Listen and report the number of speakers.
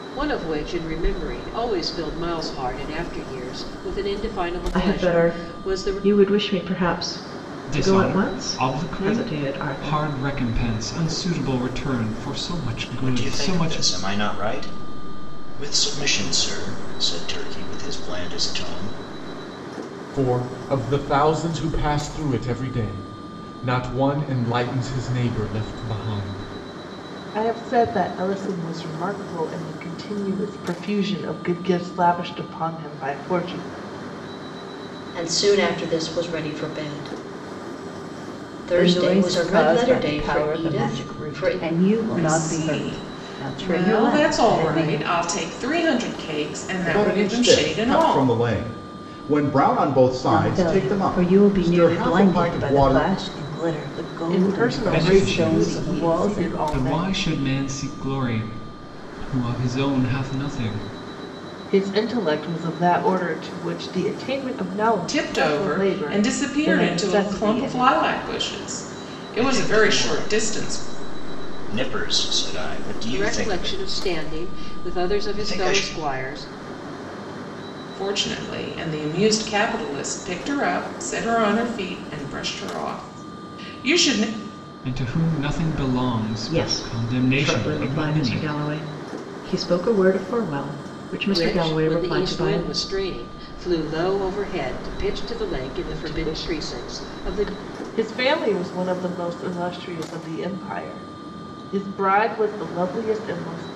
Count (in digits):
10